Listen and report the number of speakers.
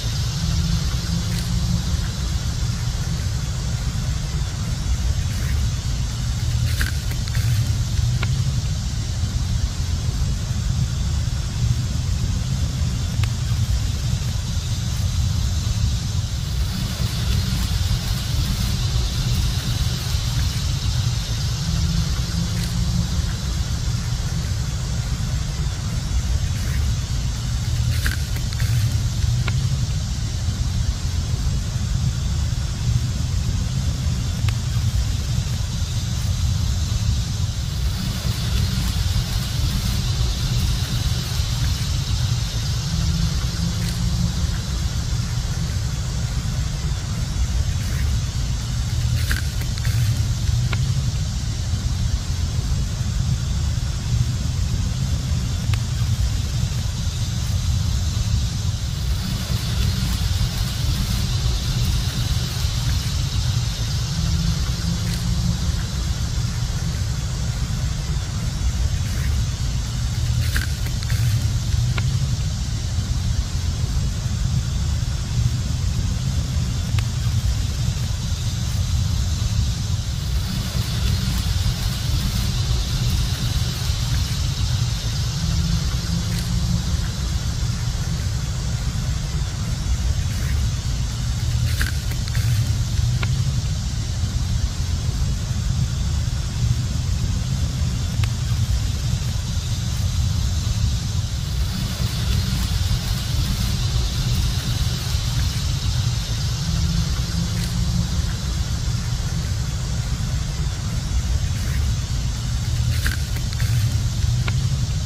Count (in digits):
0